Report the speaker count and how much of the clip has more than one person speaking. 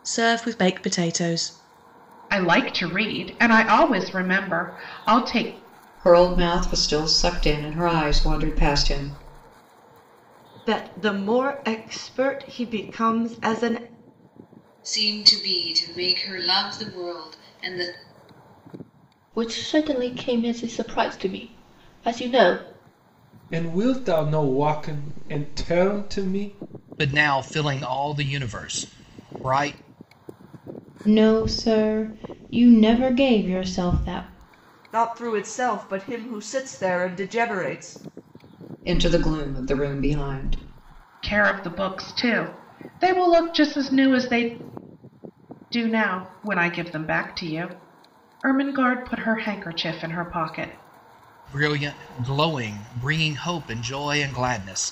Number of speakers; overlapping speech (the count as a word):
ten, no overlap